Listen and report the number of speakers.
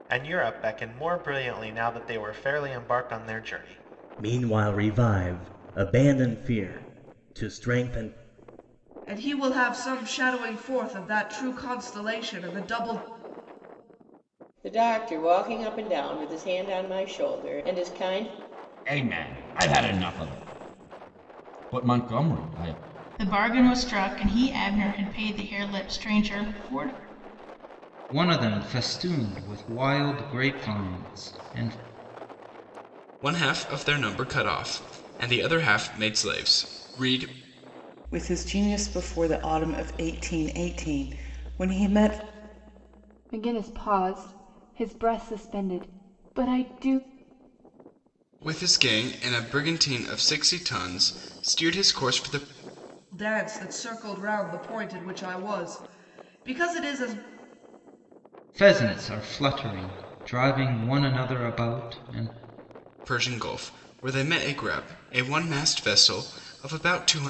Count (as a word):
ten